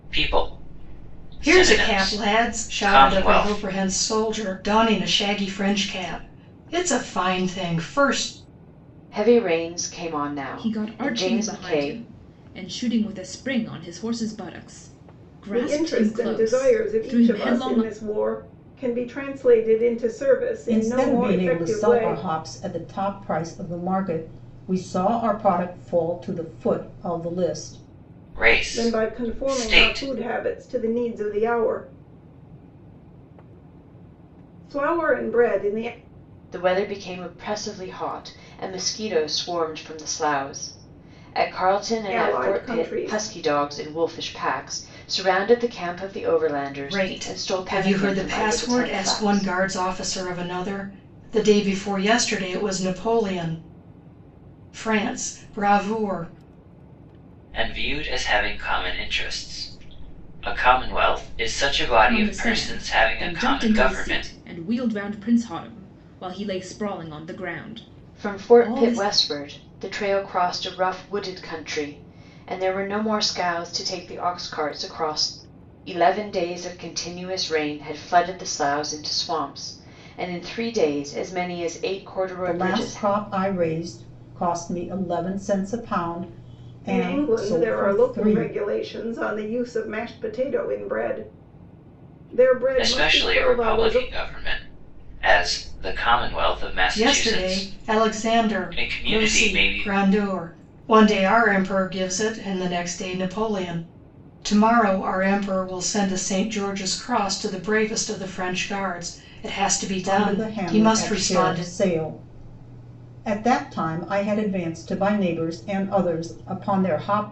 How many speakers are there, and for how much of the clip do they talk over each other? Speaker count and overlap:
six, about 21%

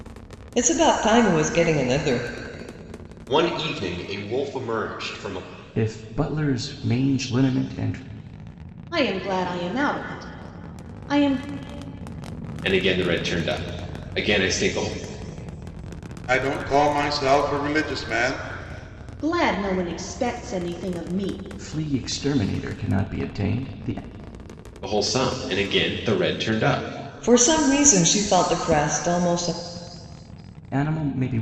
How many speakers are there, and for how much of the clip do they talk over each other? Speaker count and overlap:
six, no overlap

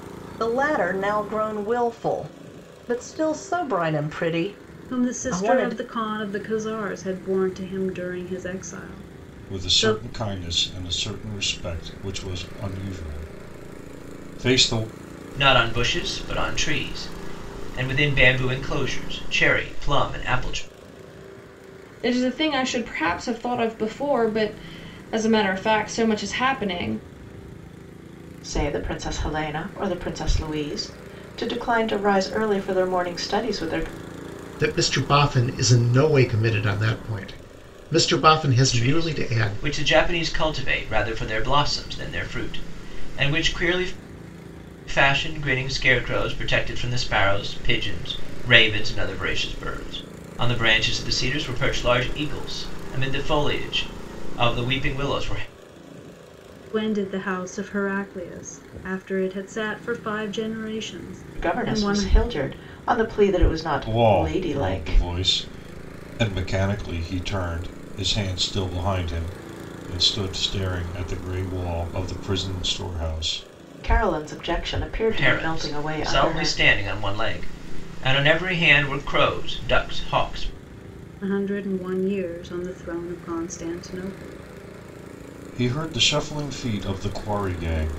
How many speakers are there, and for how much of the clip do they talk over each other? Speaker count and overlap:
seven, about 7%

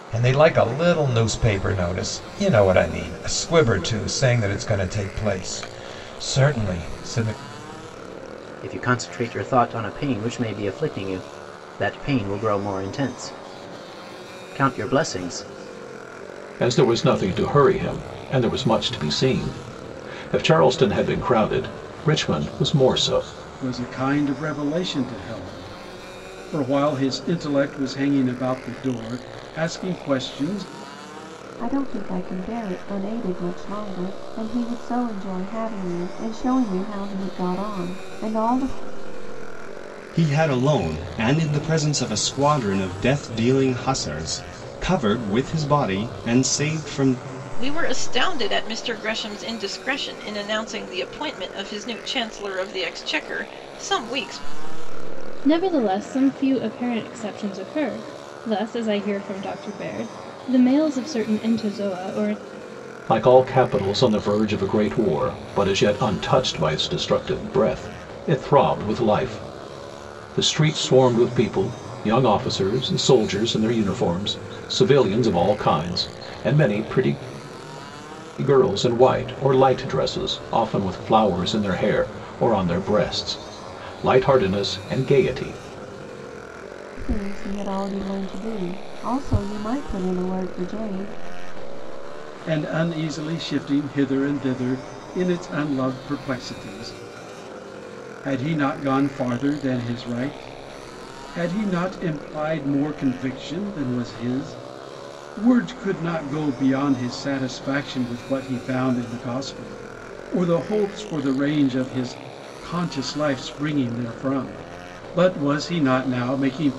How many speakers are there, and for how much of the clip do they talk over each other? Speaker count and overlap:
eight, no overlap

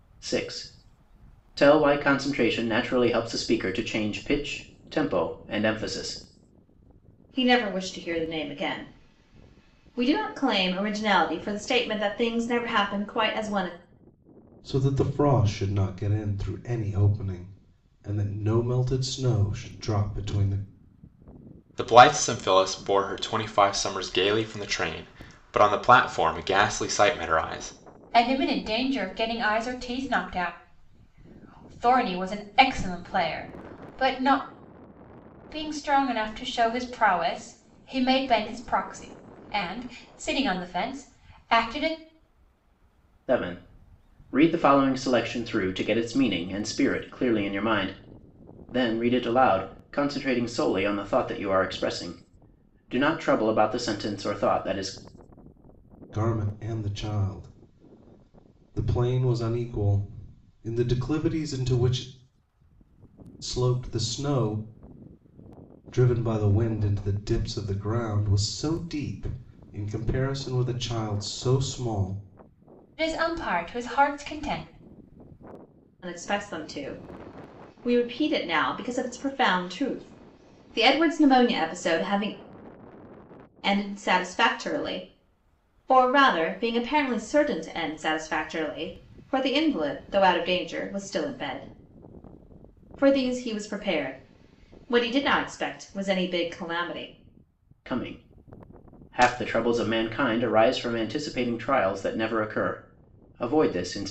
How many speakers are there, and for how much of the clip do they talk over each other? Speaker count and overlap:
five, no overlap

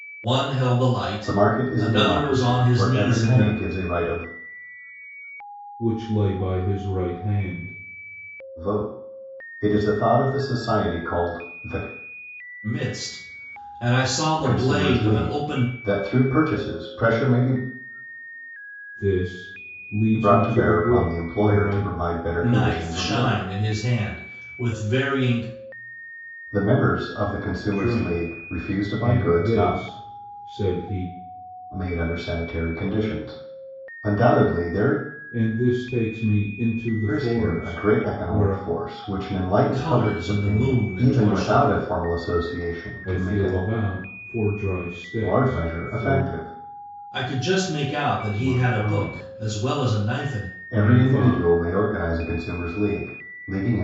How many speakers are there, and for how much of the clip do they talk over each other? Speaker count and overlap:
three, about 32%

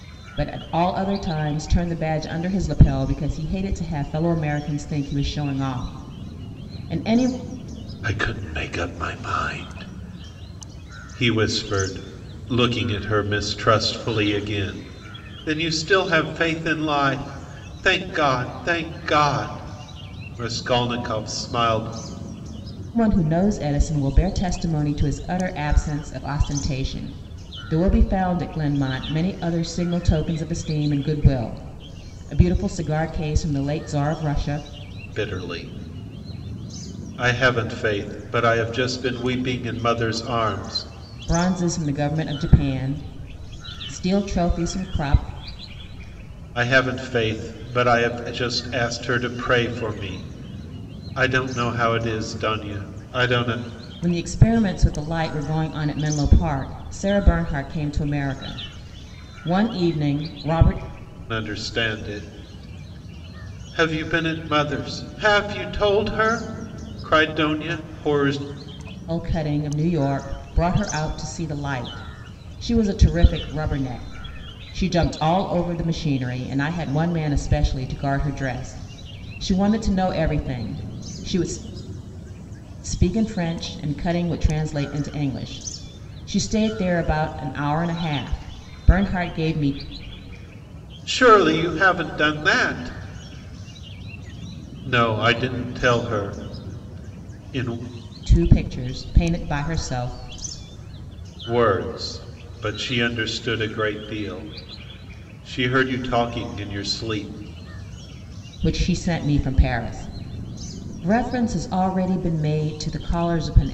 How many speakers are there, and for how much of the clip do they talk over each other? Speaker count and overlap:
two, no overlap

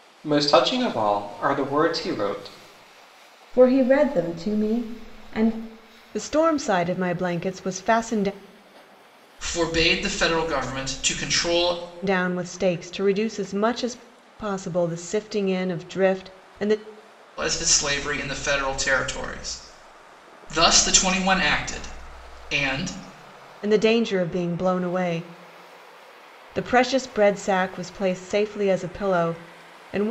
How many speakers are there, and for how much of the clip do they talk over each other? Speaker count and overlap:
four, no overlap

